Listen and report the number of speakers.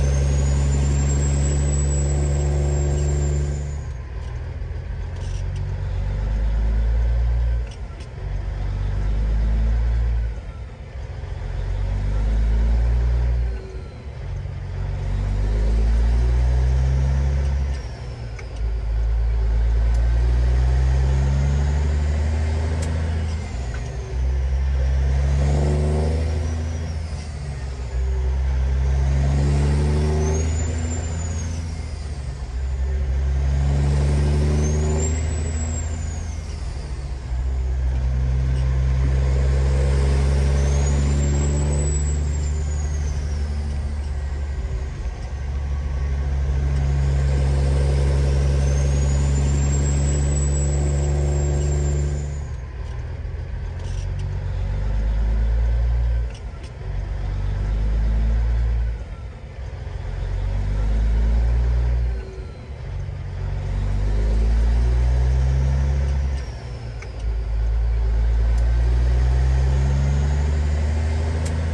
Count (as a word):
zero